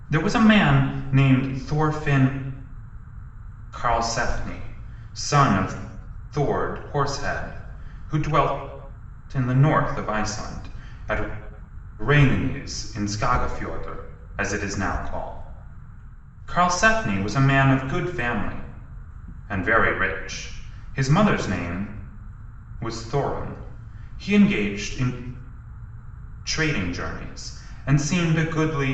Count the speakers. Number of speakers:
one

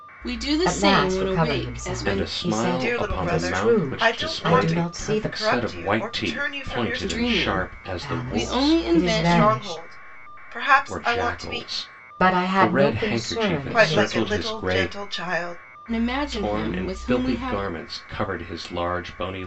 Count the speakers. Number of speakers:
four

